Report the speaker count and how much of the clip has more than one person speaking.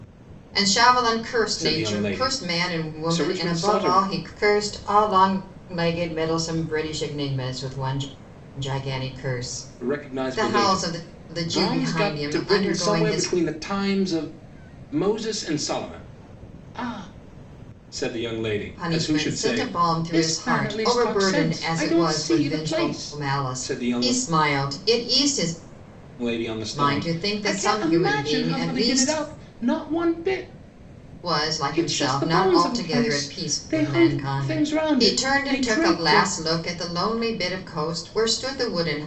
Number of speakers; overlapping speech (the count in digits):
2, about 46%